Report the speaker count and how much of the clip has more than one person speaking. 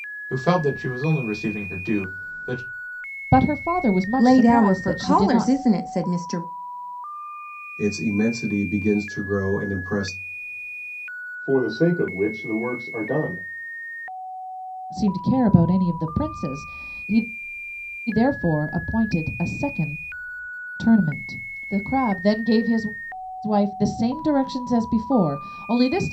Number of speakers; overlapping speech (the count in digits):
5, about 5%